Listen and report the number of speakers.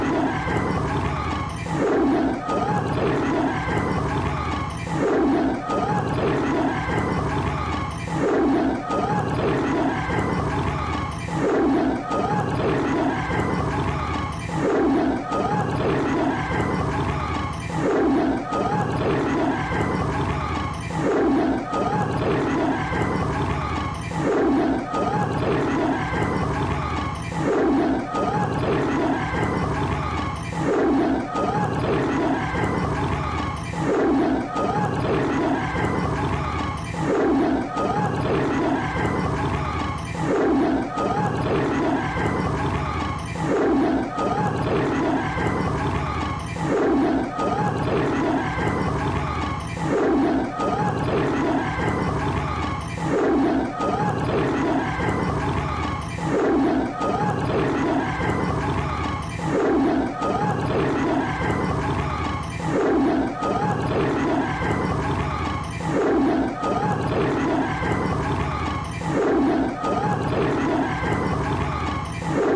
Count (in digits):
0